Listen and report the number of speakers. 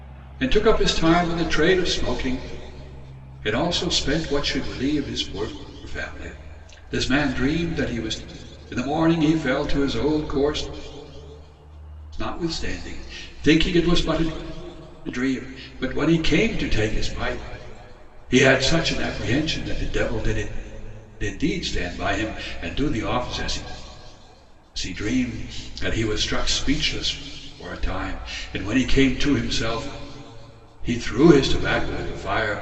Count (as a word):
one